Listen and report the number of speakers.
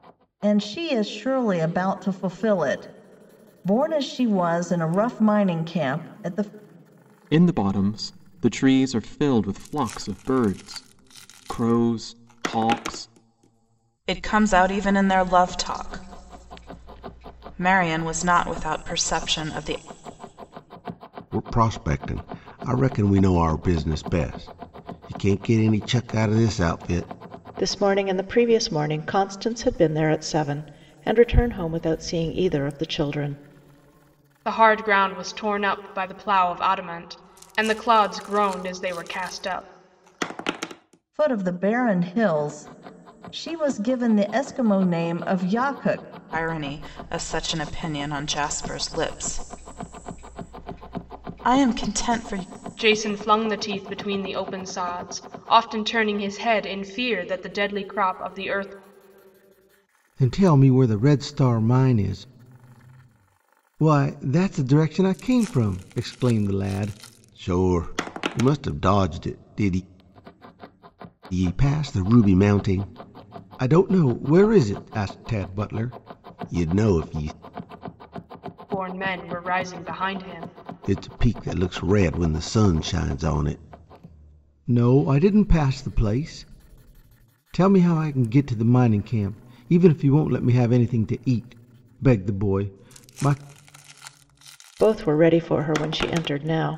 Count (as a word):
six